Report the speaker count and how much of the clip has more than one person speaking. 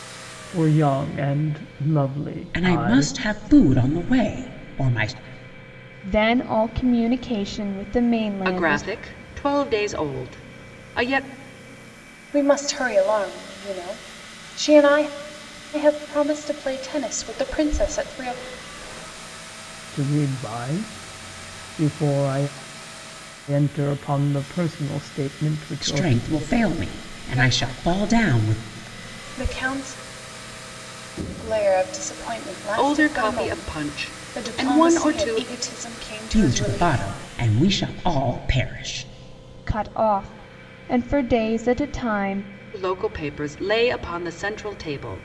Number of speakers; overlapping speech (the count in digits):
5, about 13%